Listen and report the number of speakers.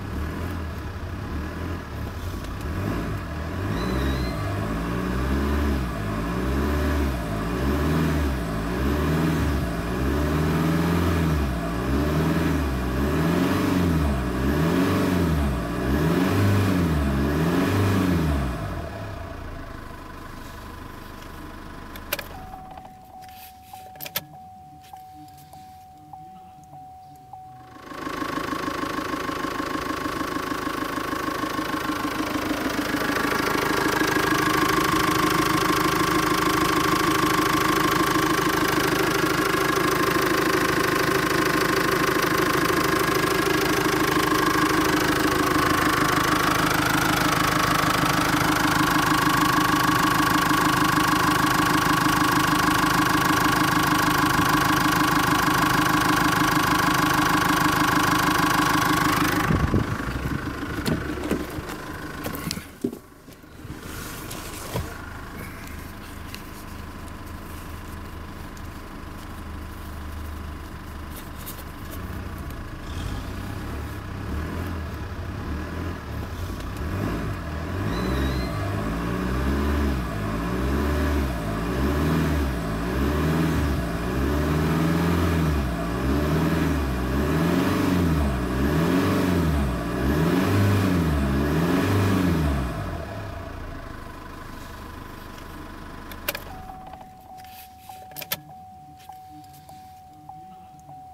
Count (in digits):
0